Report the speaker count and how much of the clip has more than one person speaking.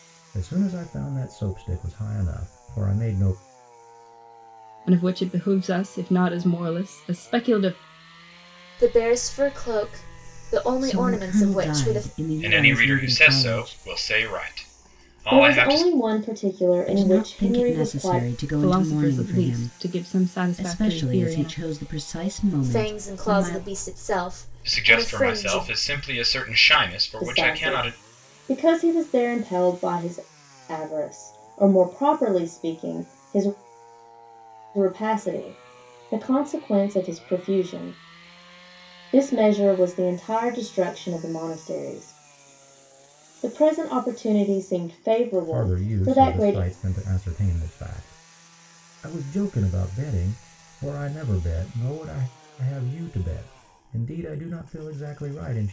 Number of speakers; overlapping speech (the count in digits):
6, about 20%